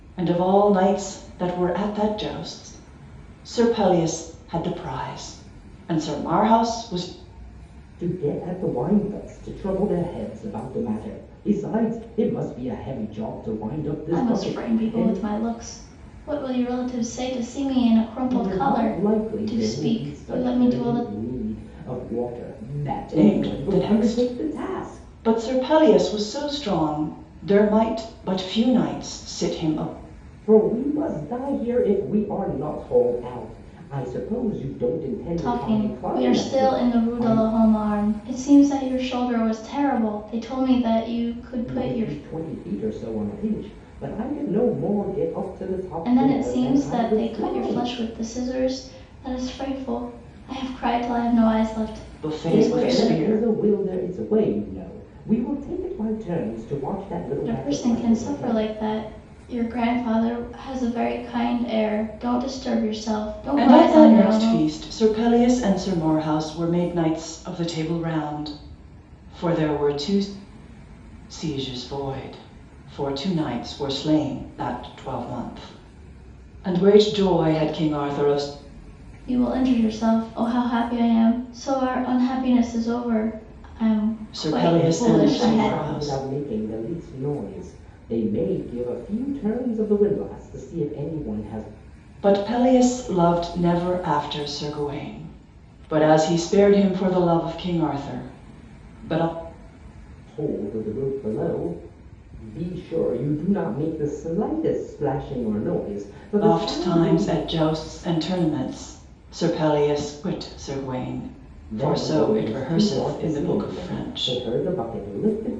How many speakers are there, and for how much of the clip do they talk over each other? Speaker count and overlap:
3, about 17%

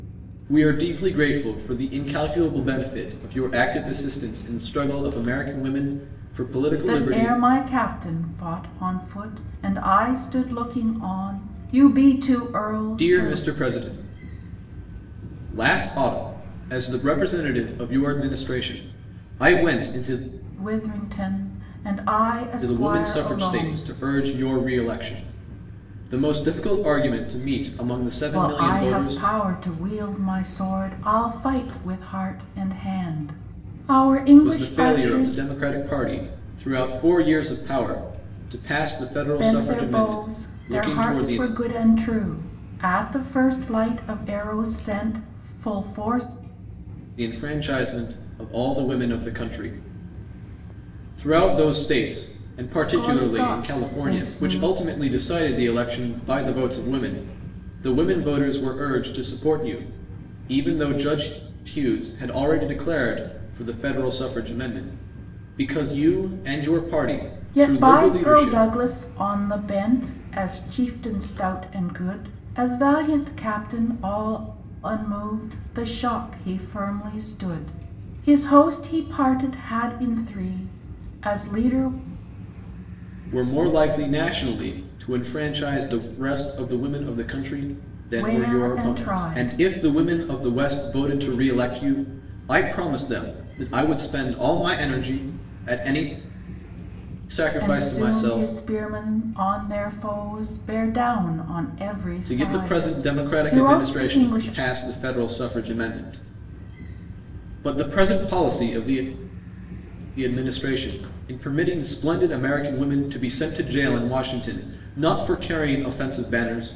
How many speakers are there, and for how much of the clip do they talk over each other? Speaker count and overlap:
2, about 12%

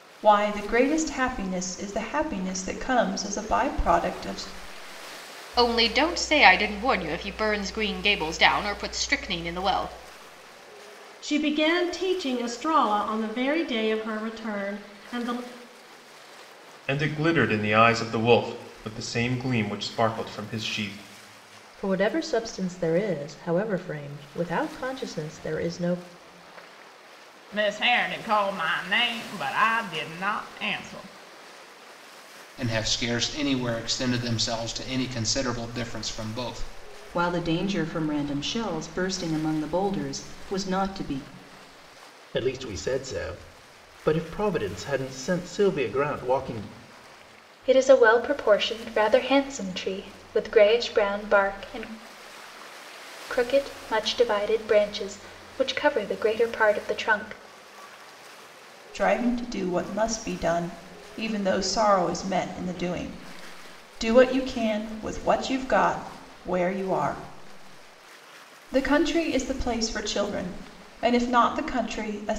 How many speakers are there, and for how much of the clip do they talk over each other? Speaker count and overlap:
10, no overlap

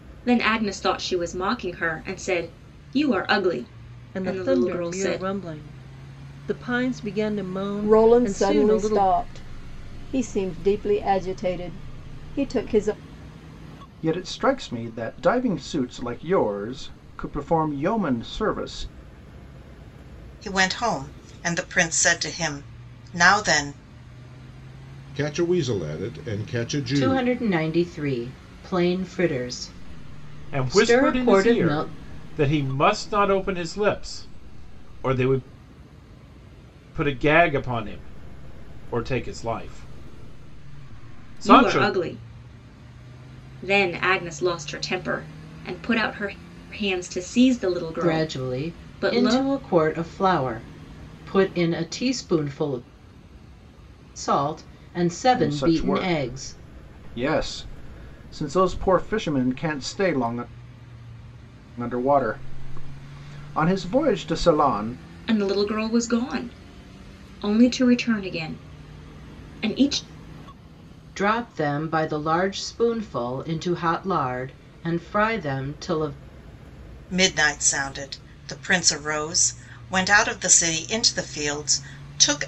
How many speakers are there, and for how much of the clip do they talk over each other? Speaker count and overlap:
8, about 9%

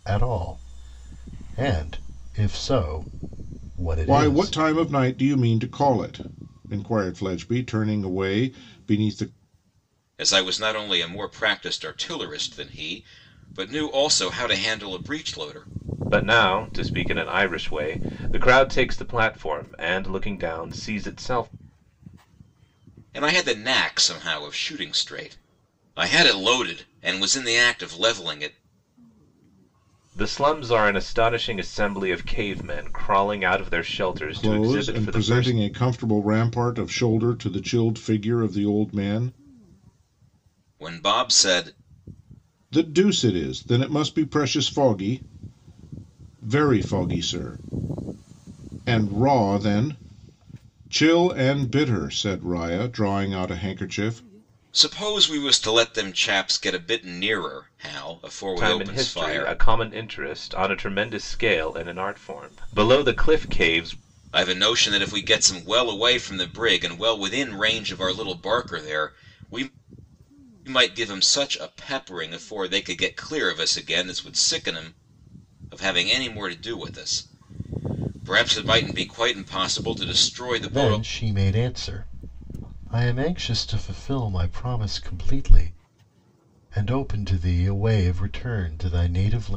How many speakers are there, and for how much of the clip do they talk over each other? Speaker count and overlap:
4, about 4%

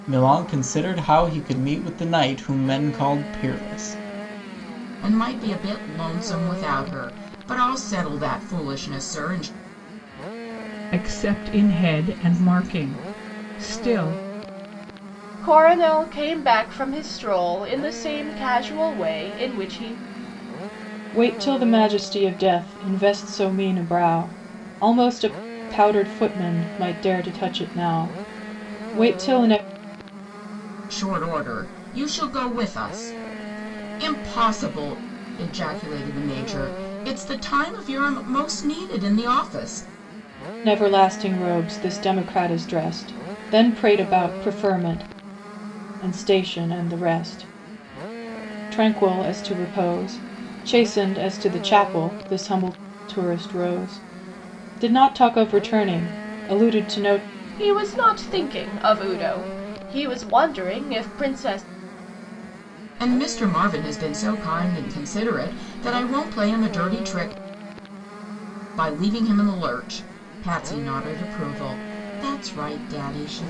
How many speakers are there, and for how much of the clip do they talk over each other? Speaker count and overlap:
5, no overlap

